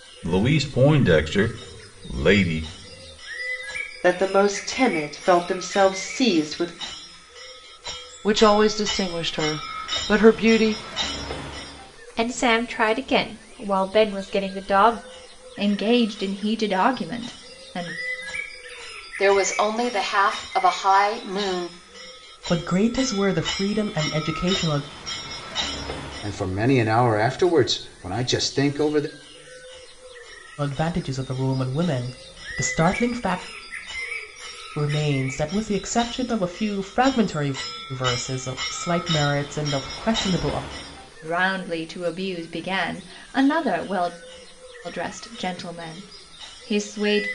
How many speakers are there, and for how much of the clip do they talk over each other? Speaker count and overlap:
eight, no overlap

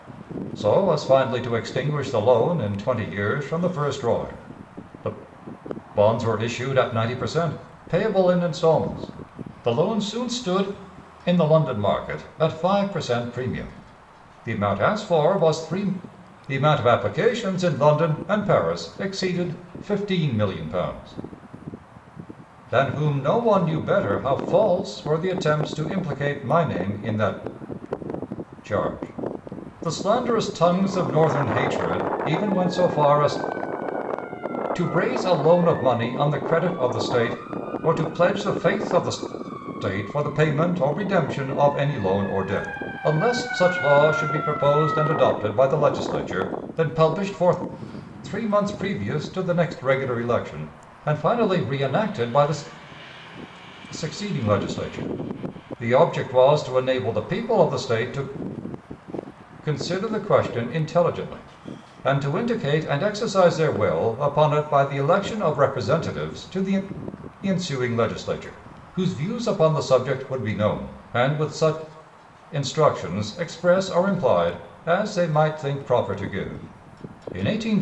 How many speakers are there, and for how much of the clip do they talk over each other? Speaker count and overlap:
one, no overlap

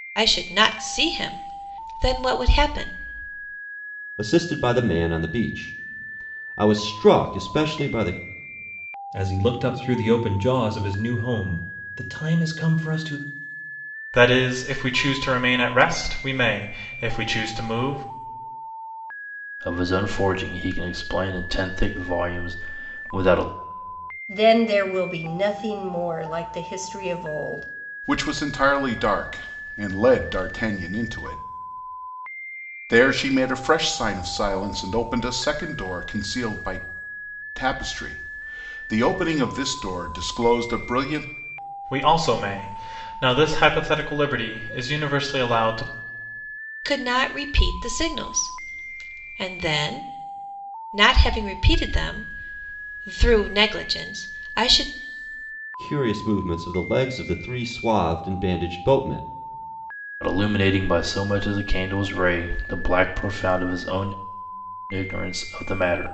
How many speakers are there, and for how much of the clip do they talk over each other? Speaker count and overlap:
seven, no overlap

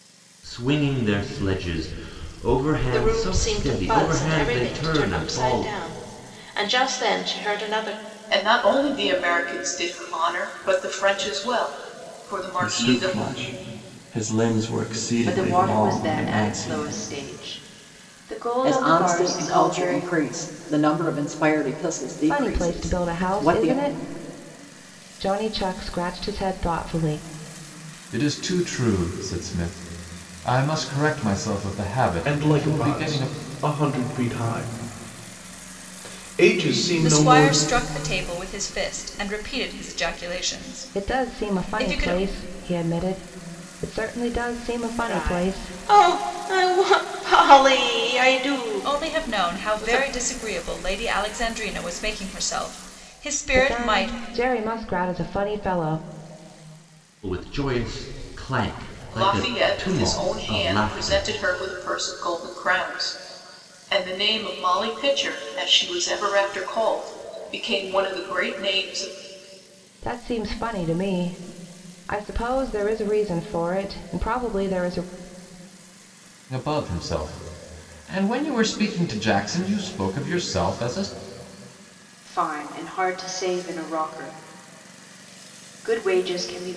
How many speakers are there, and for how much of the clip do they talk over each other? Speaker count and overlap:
ten, about 19%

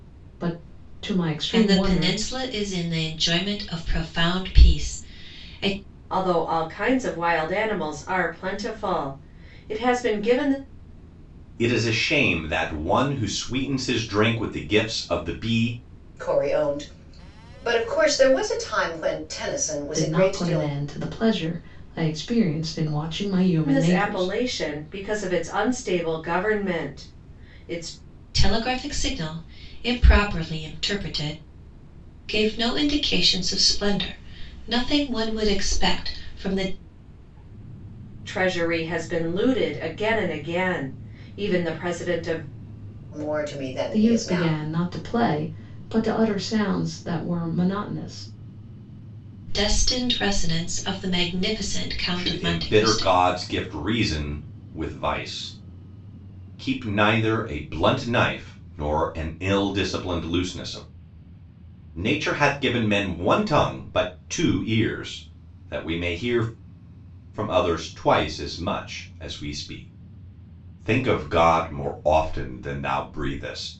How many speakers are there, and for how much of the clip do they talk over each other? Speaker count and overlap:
five, about 5%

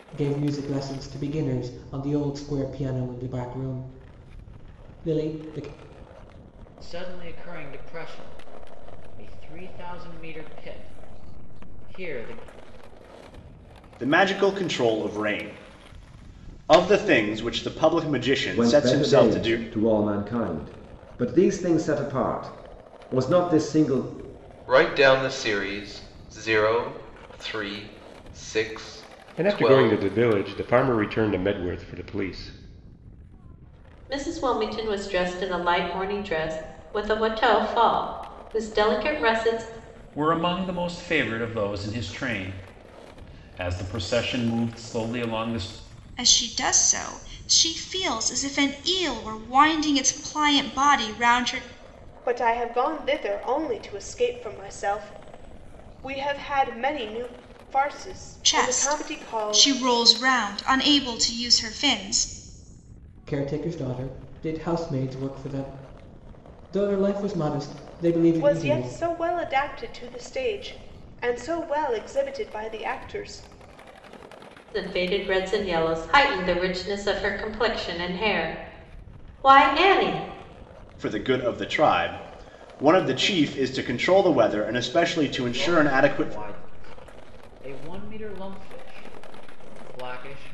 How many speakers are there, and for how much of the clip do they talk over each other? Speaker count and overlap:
ten, about 5%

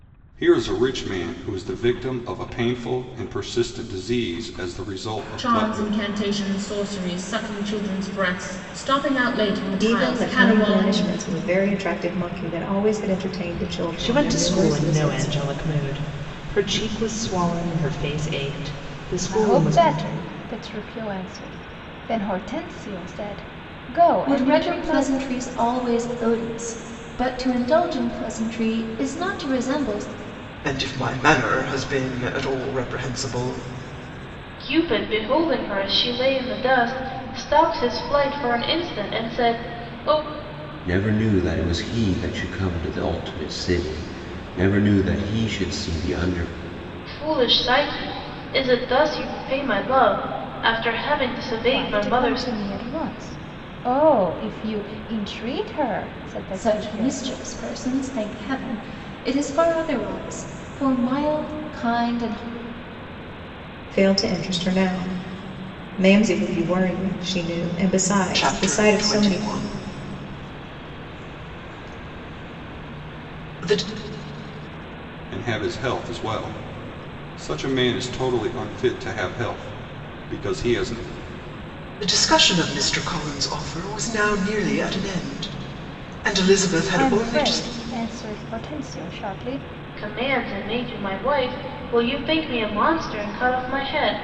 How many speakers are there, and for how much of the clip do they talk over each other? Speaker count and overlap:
nine, about 9%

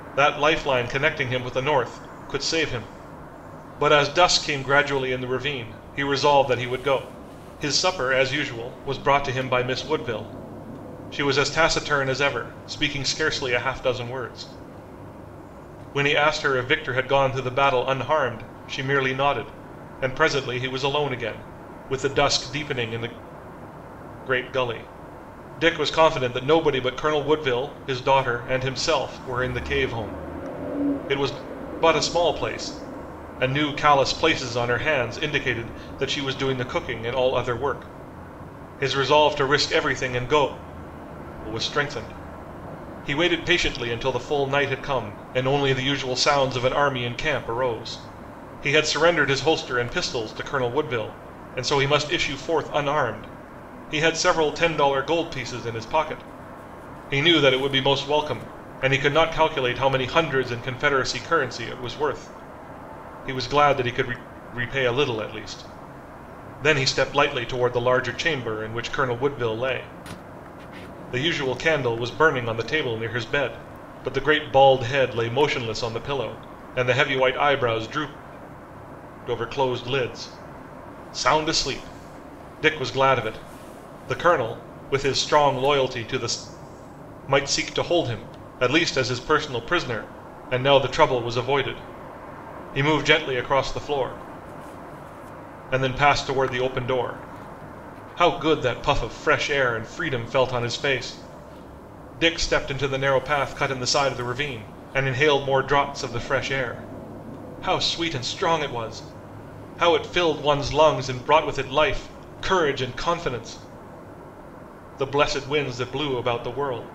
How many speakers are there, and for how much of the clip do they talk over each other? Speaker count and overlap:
one, no overlap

